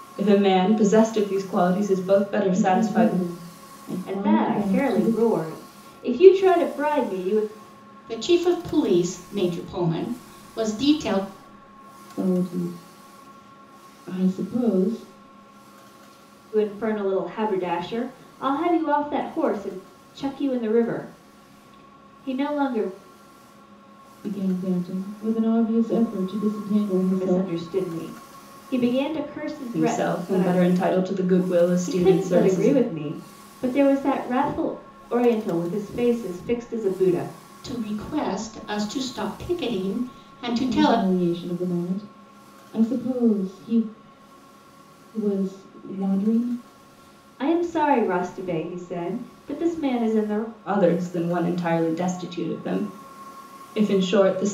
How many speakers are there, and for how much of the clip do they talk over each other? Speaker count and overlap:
4, about 9%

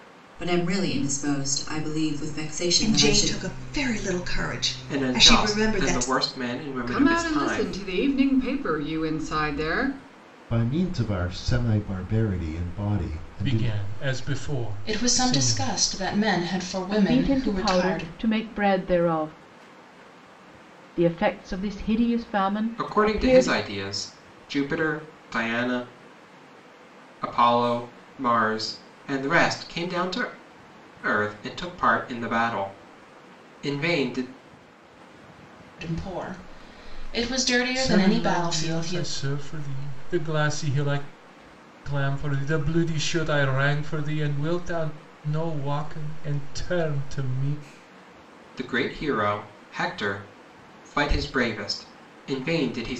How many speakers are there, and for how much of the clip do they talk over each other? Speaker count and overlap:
8, about 14%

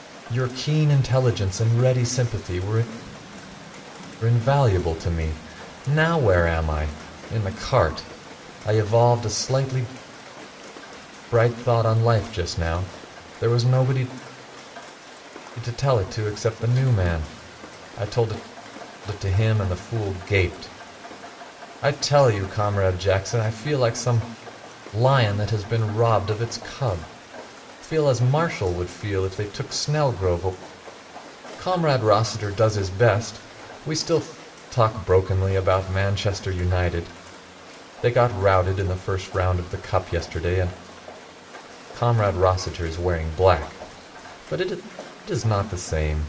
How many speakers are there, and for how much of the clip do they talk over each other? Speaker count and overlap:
1, no overlap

